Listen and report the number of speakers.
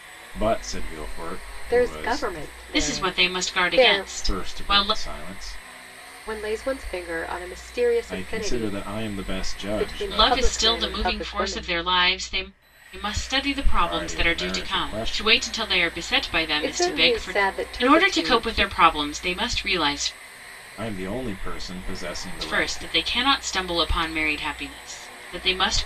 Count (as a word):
three